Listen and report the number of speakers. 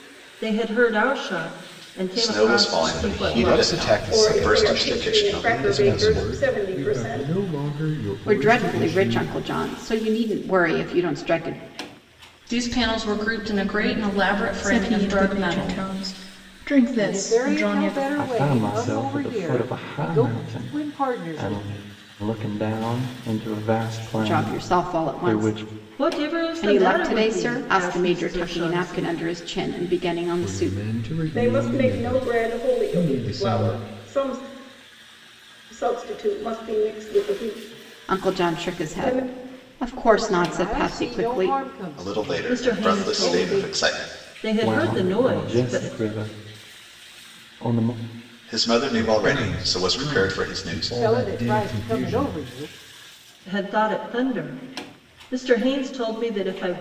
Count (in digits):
10